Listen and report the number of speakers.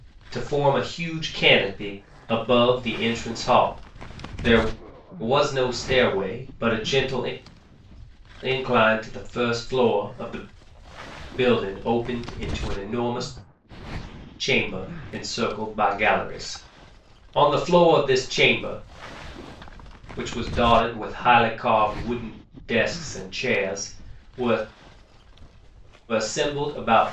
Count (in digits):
1